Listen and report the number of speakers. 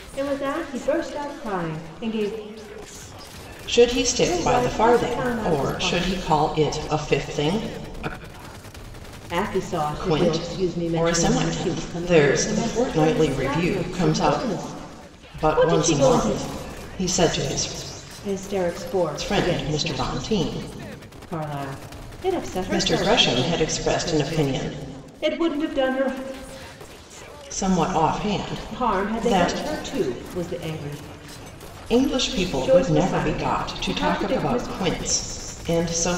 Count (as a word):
two